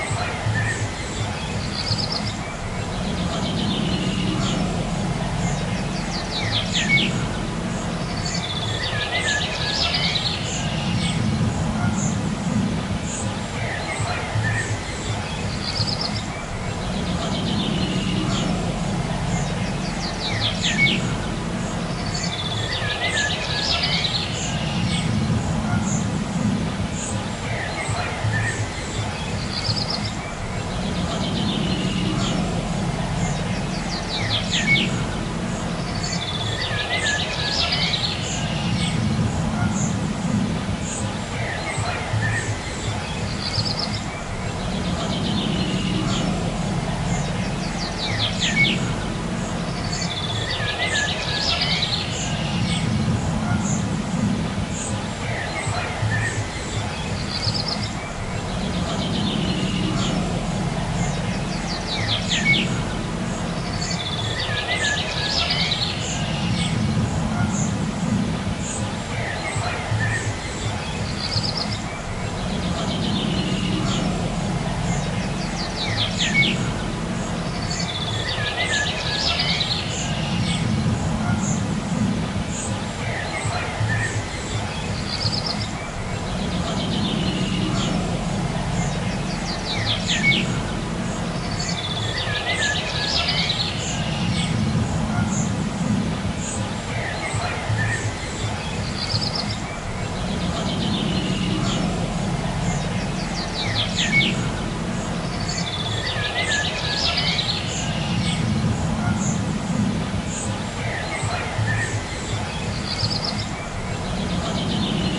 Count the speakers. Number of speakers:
0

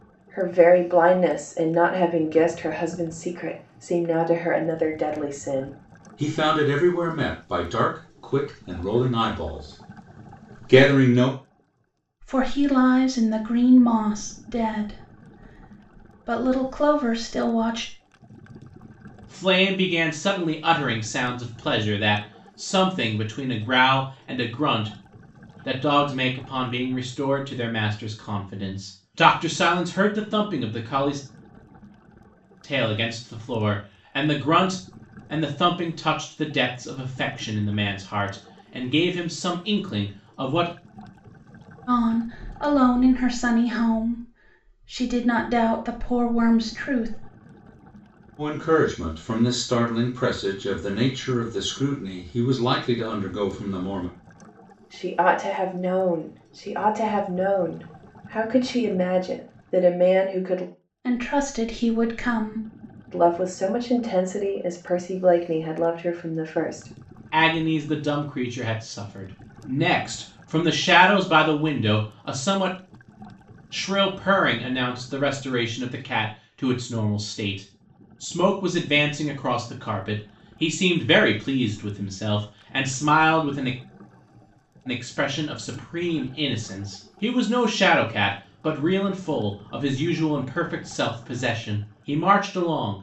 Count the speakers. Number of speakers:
4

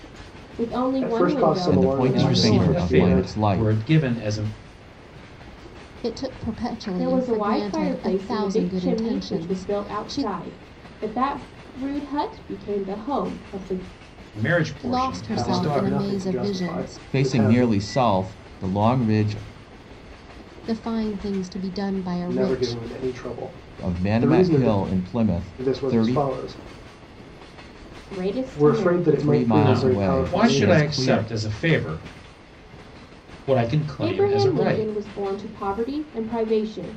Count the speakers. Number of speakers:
5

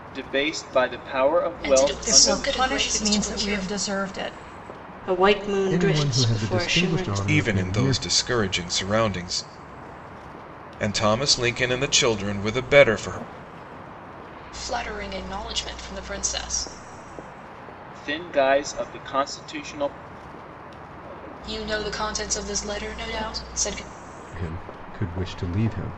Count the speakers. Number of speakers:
6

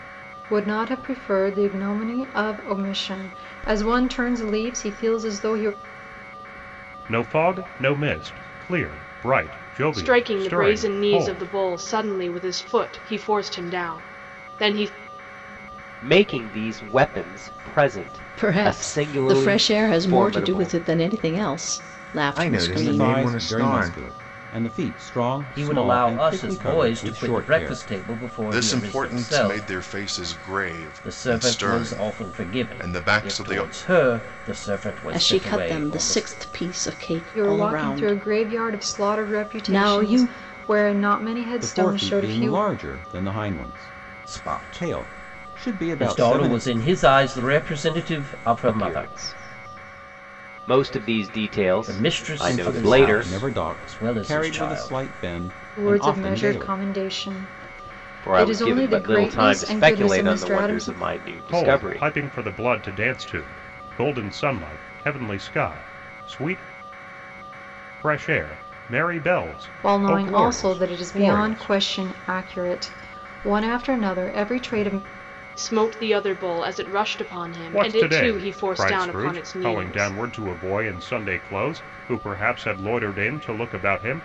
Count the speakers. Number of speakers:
9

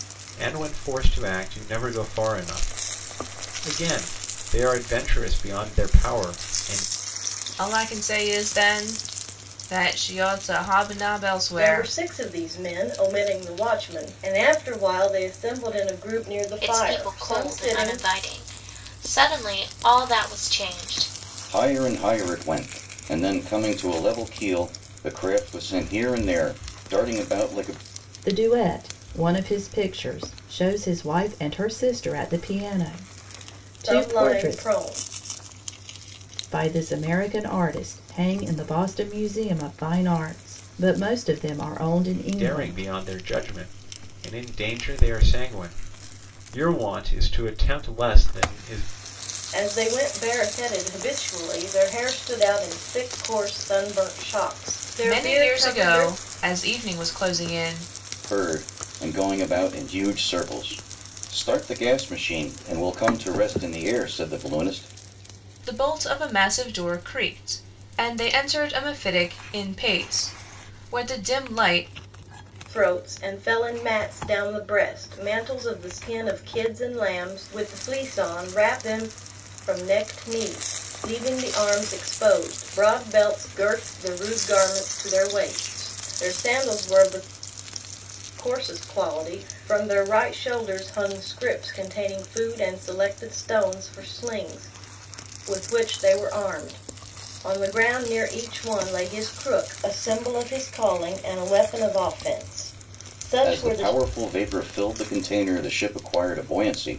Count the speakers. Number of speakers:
6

